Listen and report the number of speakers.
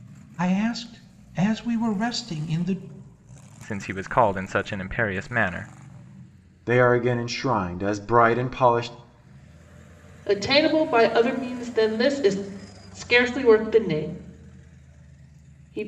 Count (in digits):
4